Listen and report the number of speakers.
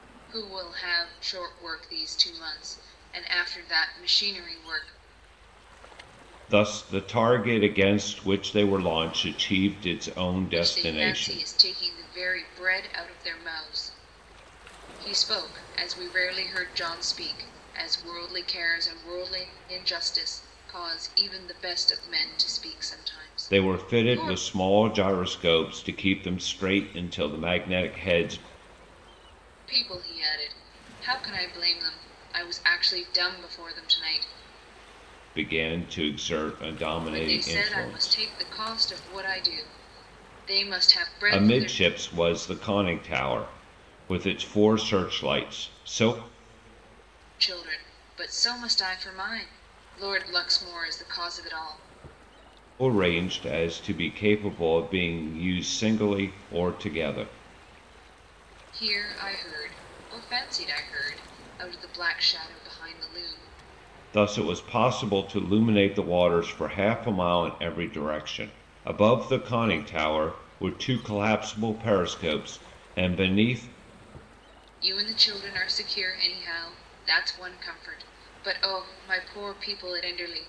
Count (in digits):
2